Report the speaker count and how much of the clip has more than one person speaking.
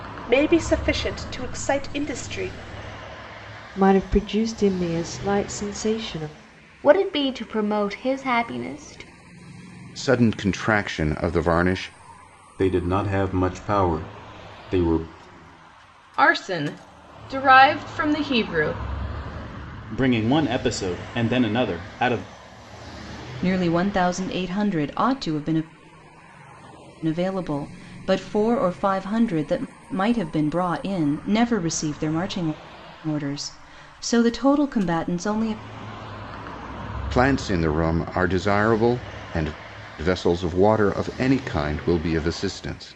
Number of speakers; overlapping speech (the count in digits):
8, no overlap